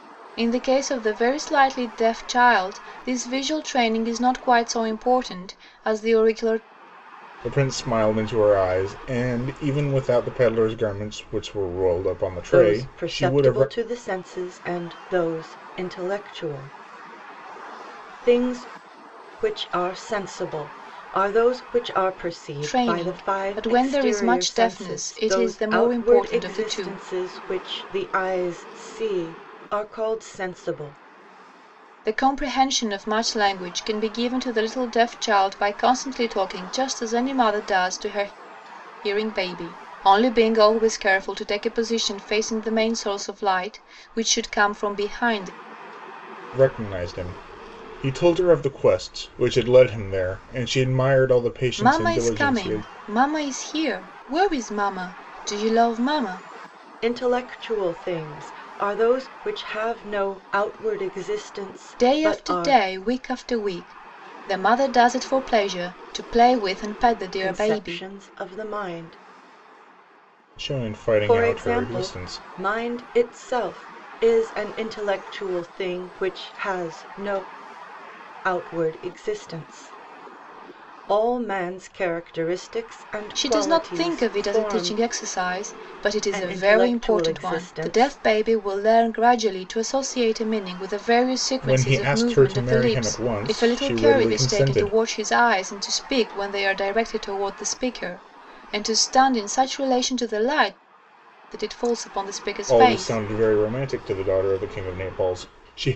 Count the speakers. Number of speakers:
three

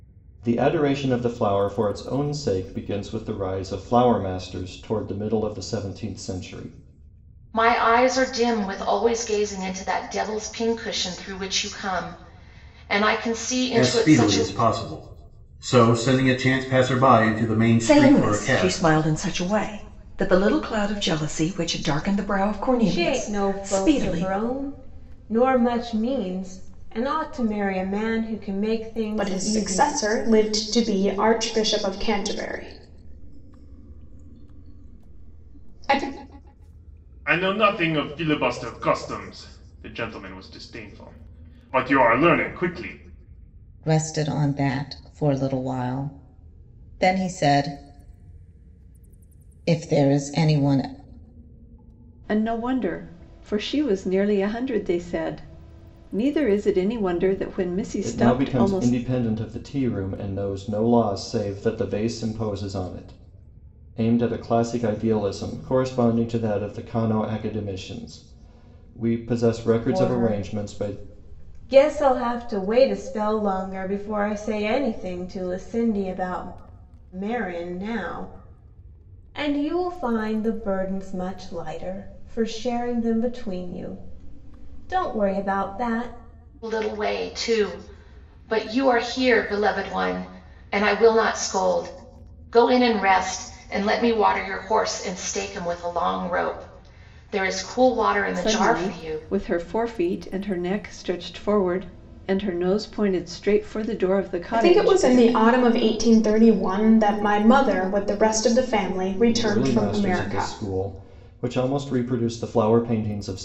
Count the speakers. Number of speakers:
nine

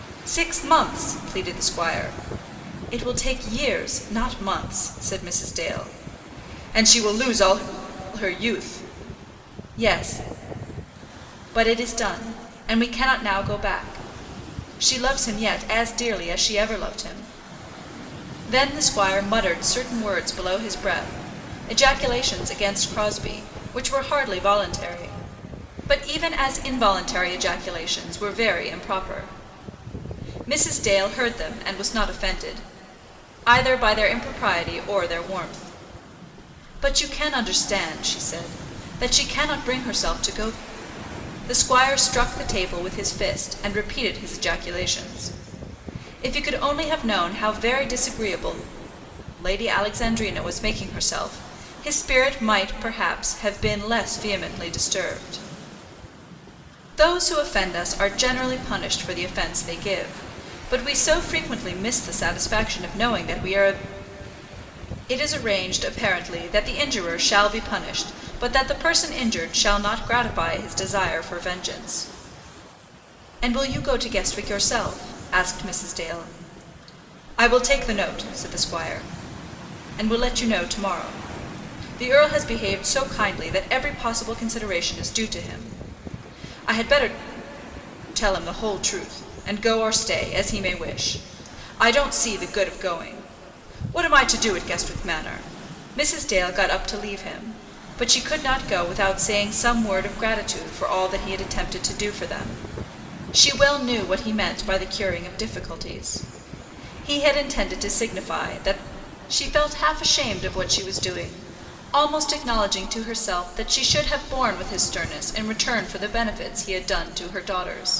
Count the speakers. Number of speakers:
one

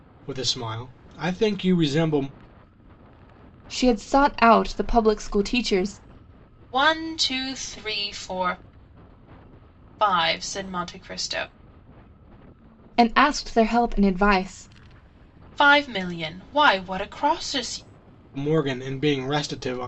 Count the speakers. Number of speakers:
three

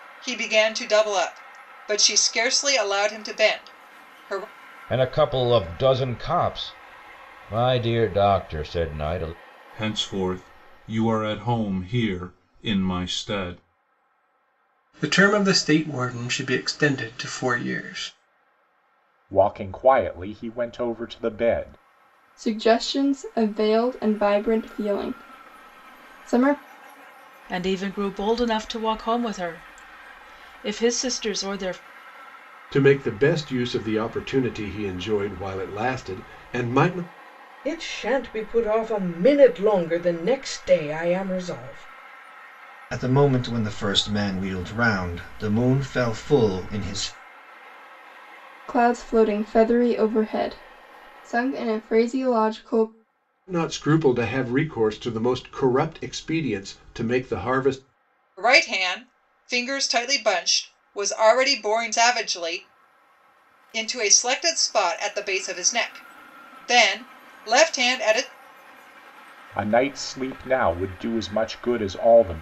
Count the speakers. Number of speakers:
ten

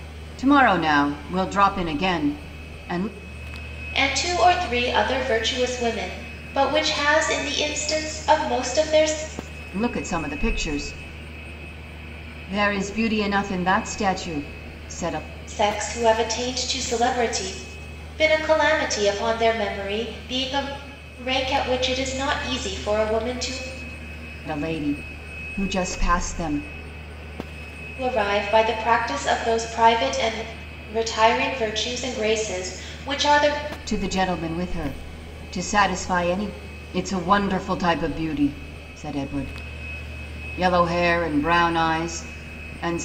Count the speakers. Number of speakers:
two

